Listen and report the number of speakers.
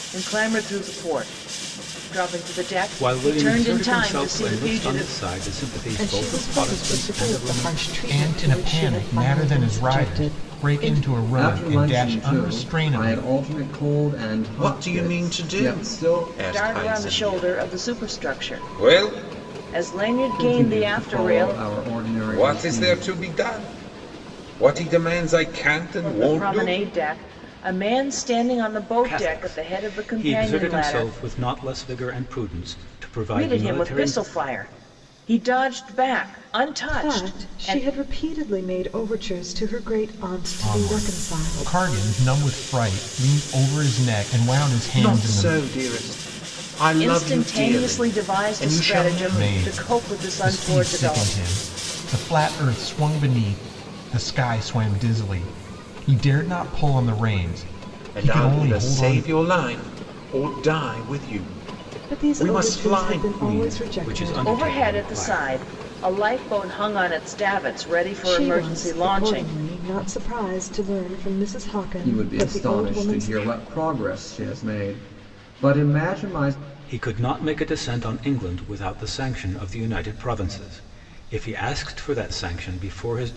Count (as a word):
six